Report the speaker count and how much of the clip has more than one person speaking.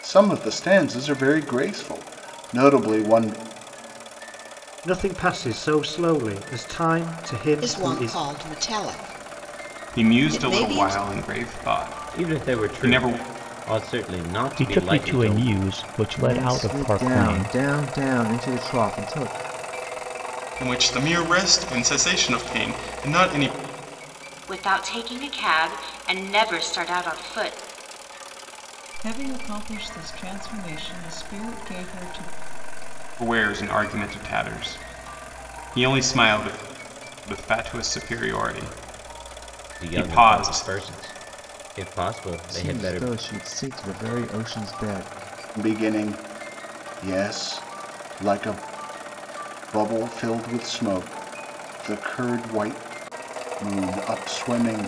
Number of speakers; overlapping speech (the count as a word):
ten, about 13%